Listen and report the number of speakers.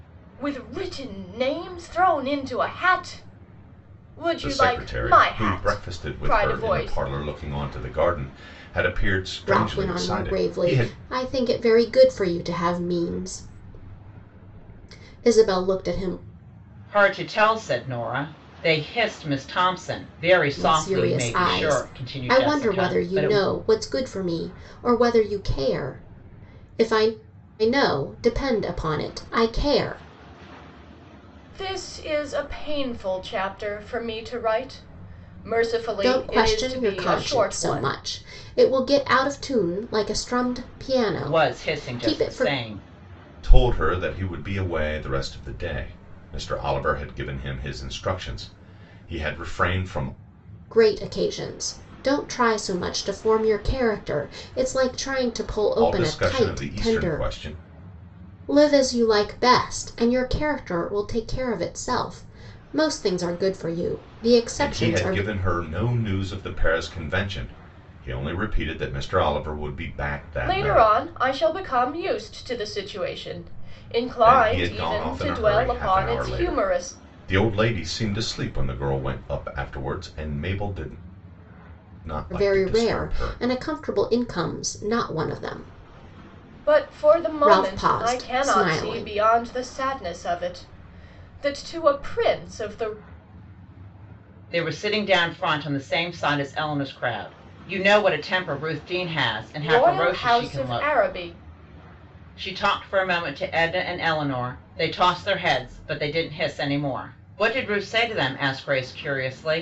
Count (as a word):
four